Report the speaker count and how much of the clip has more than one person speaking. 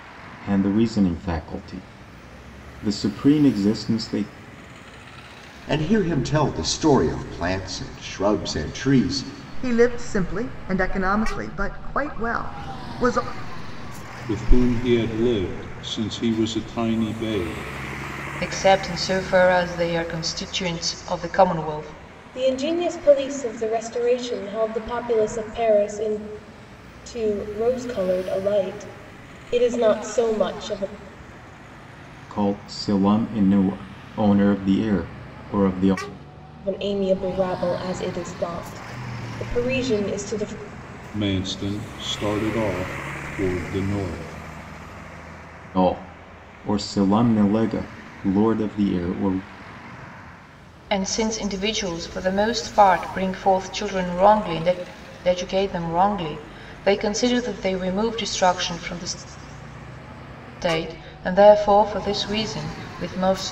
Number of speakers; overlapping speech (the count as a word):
six, no overlap